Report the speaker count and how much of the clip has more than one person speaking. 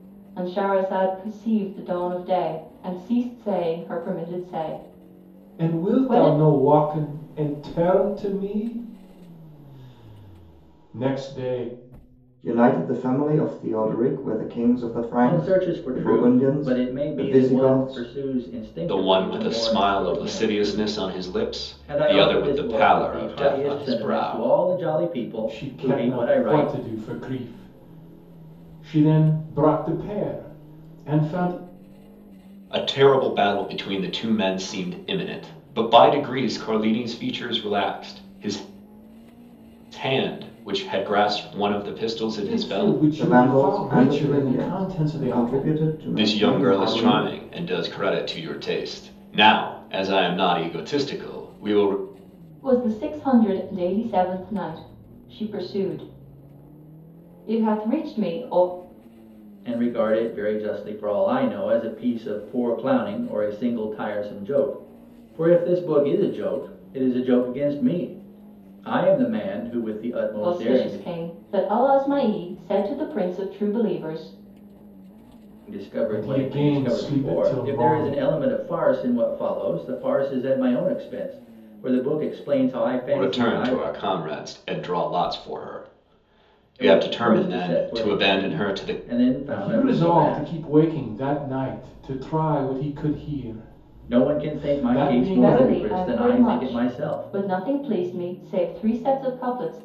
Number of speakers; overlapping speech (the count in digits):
5, about 25%